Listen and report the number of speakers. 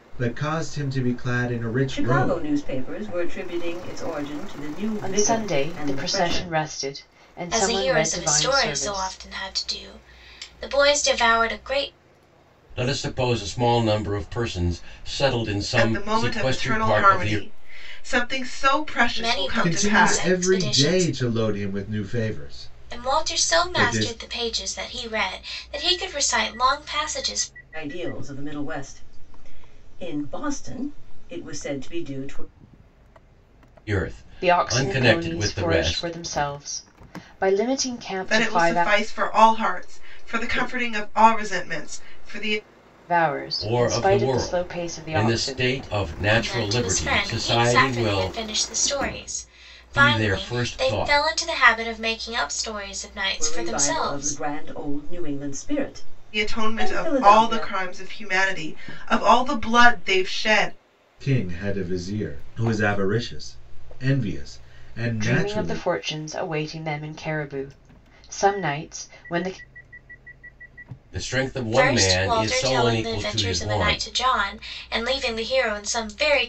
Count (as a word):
six